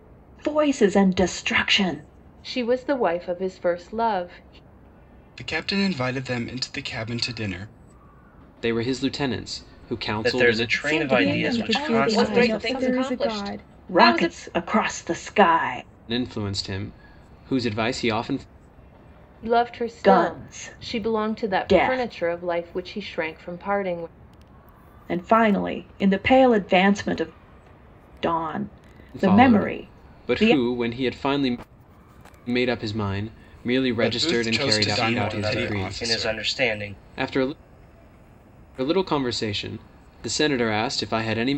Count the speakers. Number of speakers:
8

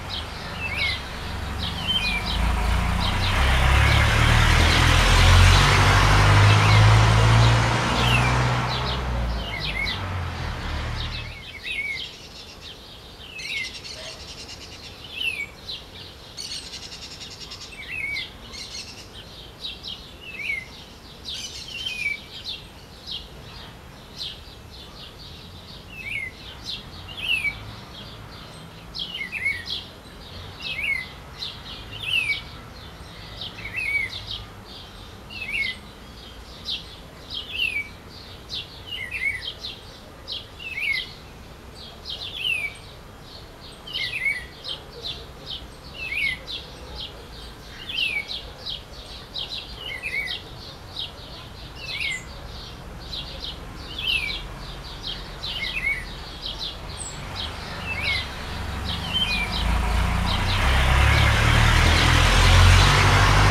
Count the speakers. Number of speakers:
0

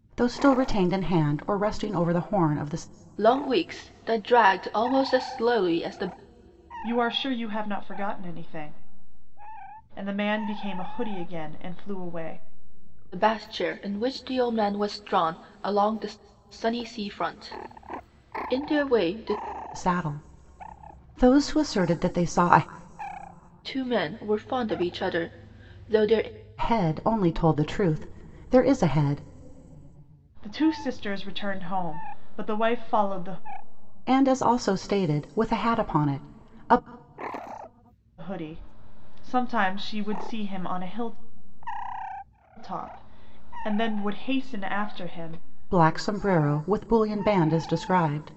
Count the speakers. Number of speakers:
3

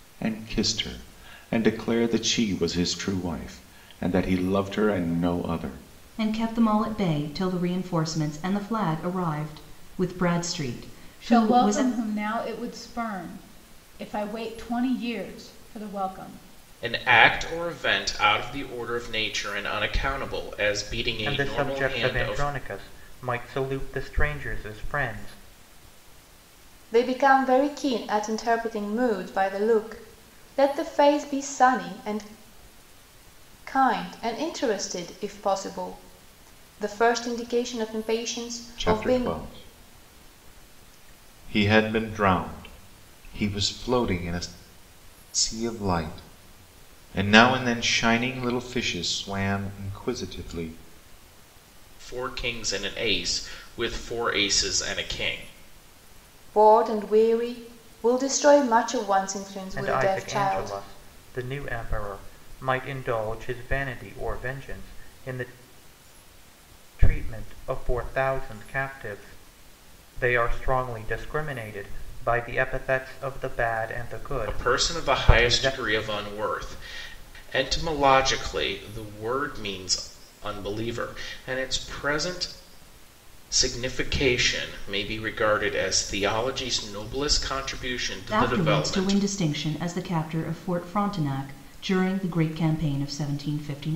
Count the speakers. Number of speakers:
6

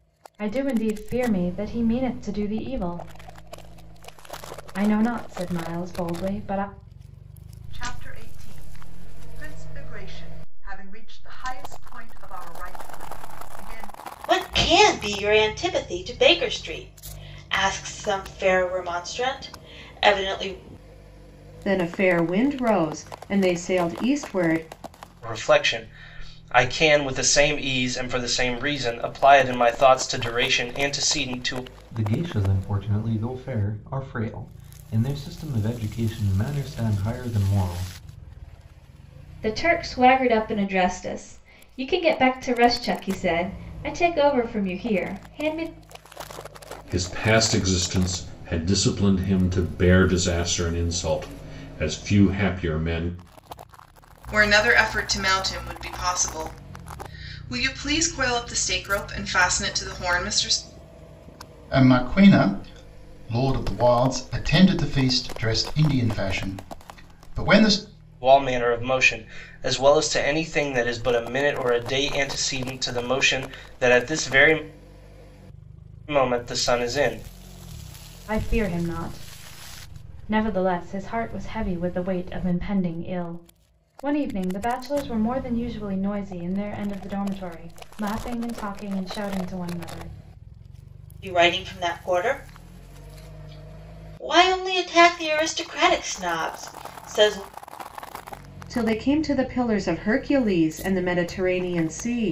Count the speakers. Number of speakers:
10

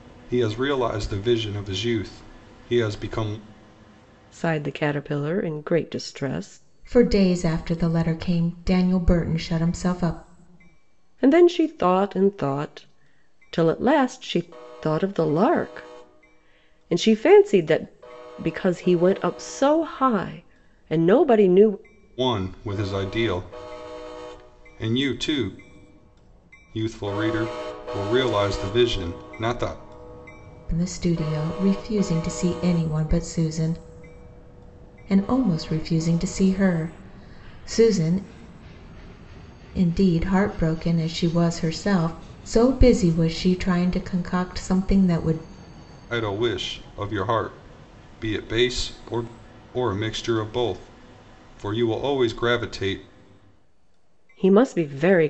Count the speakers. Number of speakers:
3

